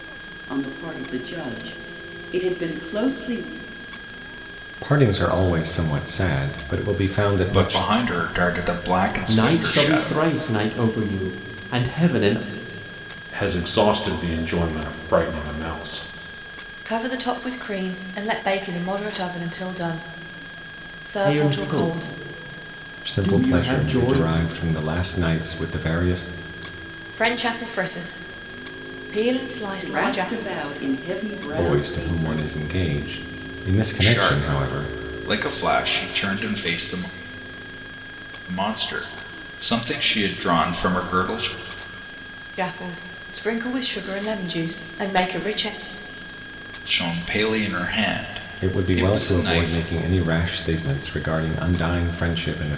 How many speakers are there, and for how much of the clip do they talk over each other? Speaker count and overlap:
6, about 14%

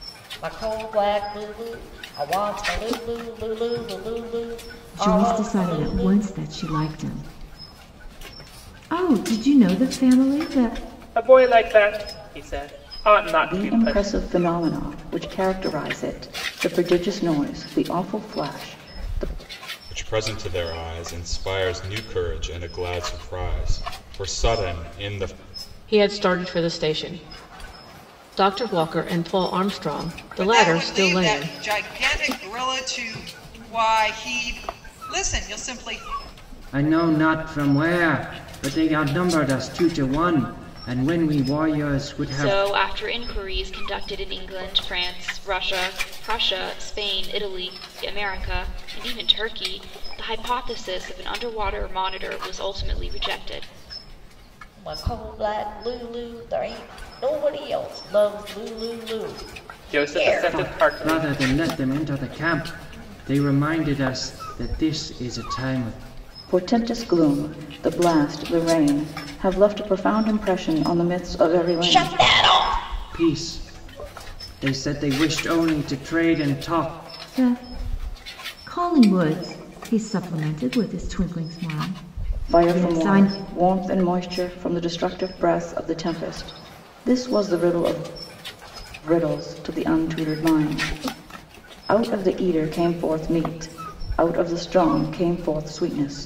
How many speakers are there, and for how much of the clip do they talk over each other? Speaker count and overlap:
9, about 7%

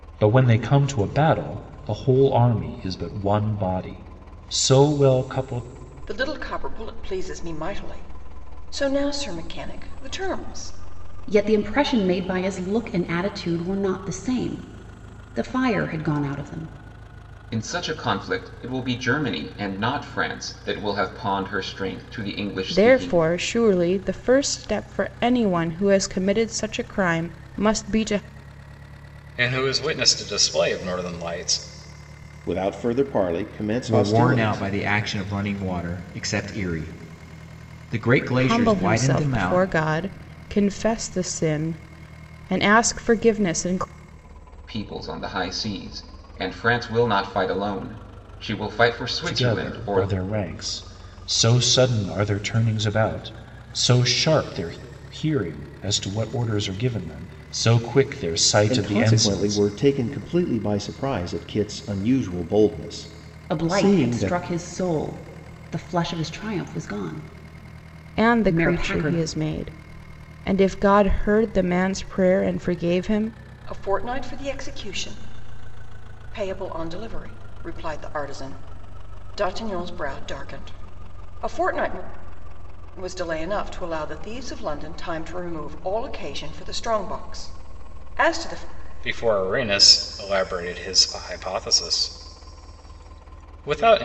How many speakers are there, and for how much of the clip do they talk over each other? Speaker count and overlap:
8, about 7%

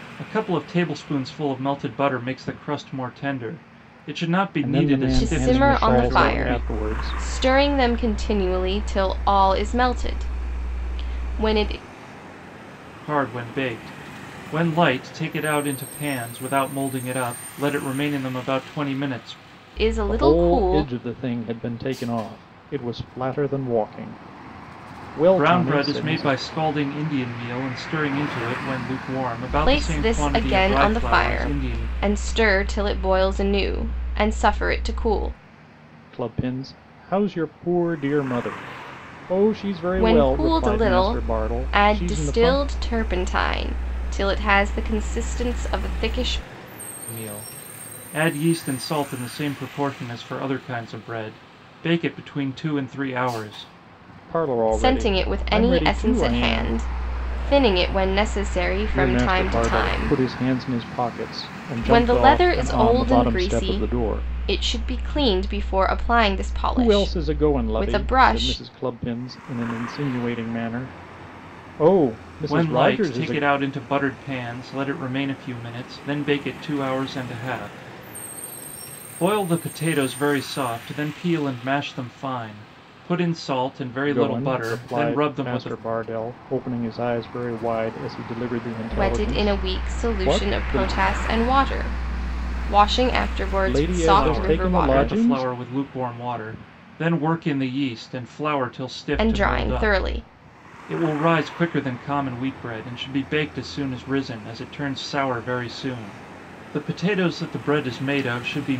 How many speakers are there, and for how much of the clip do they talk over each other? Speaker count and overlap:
3, about 23%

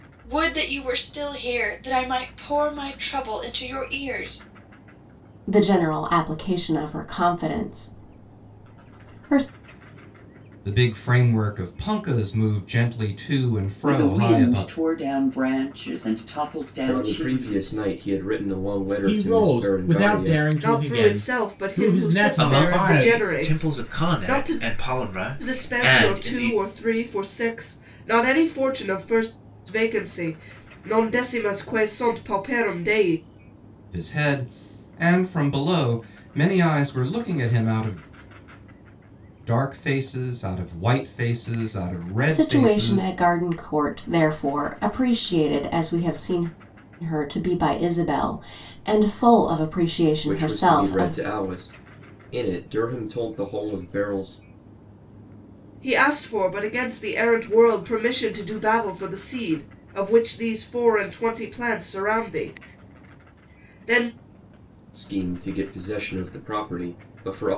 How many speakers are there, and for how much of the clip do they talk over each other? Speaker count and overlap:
8, about 15%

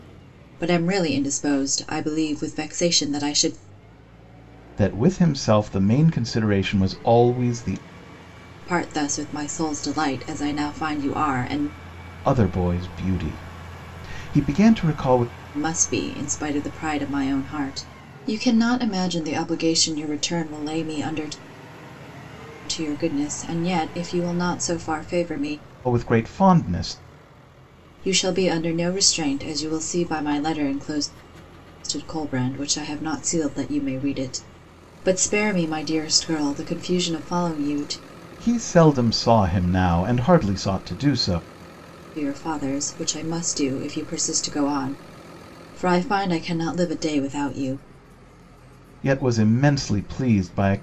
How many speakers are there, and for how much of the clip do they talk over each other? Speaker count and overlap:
2, no overlap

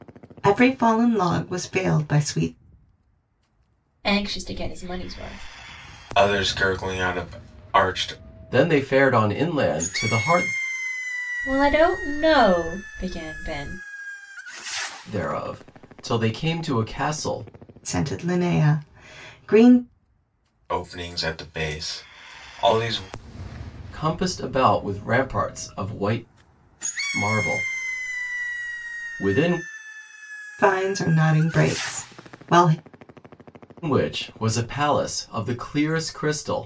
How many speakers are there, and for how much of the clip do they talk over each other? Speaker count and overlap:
4, no overlap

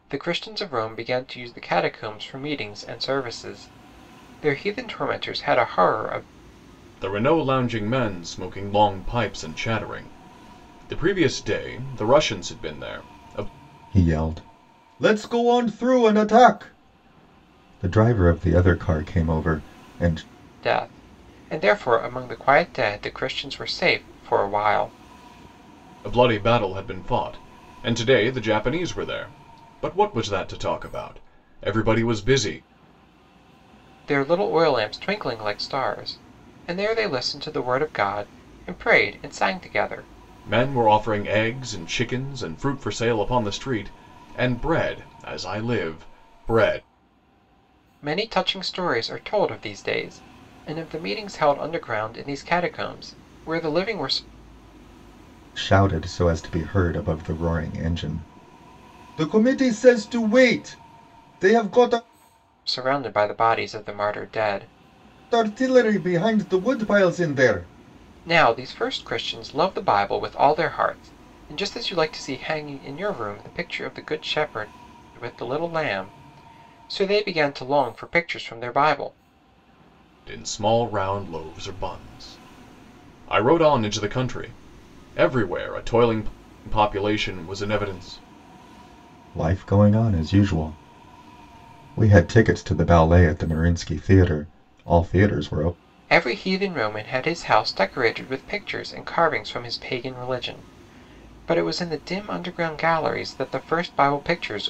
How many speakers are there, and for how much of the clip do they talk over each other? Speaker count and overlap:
3, no overlap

